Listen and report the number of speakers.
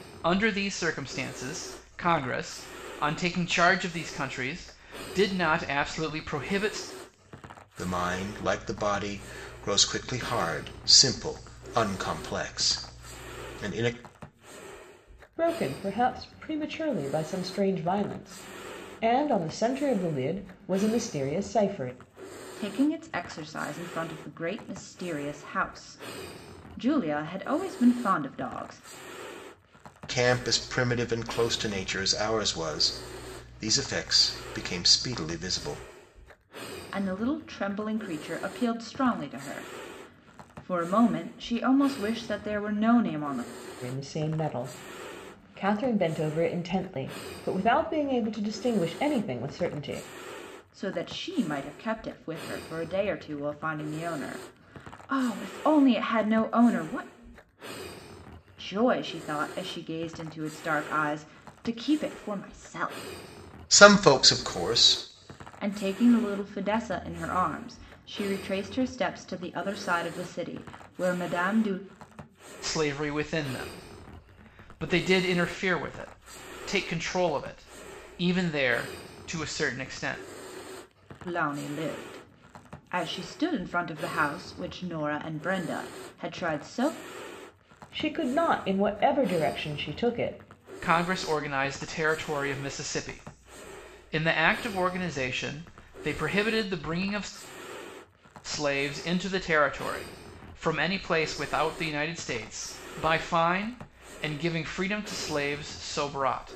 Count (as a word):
four